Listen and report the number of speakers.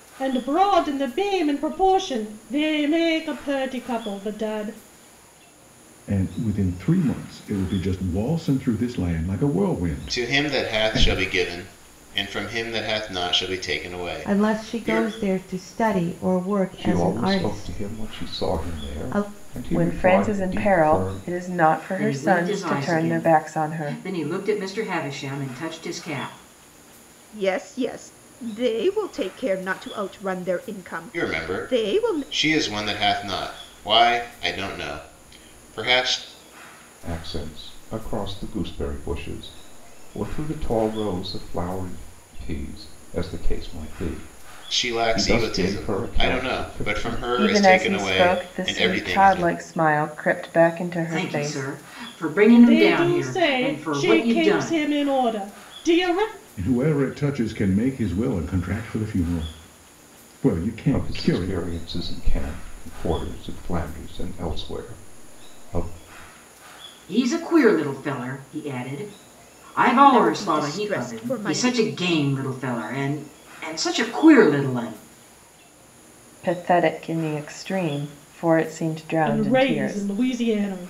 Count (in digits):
8